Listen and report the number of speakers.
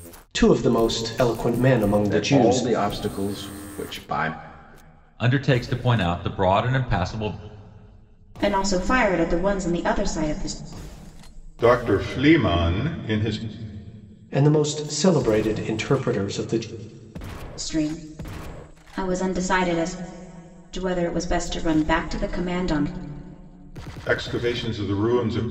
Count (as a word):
five